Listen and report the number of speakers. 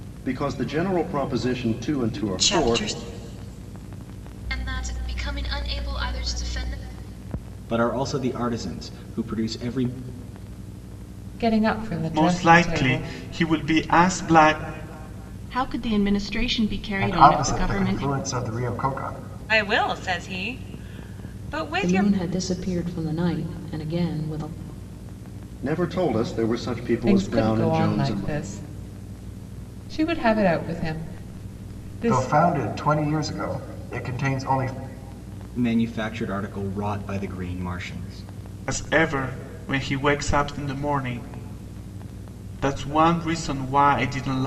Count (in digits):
10